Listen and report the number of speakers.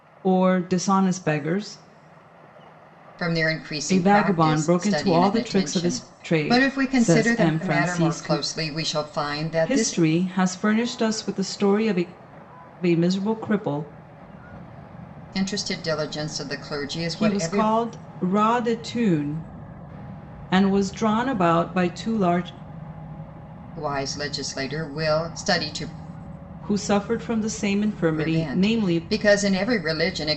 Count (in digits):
2